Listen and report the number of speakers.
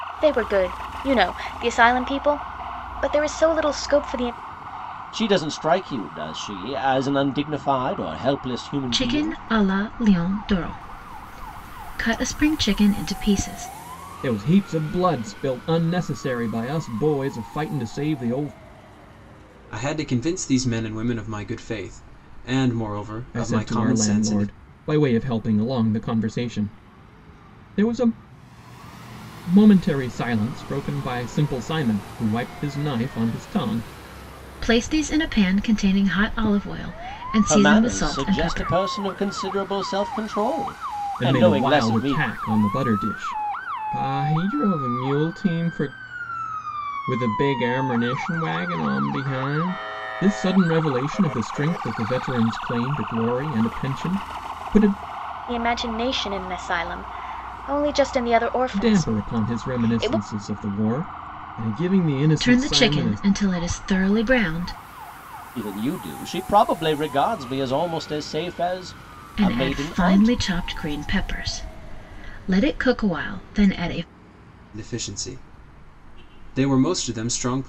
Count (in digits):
5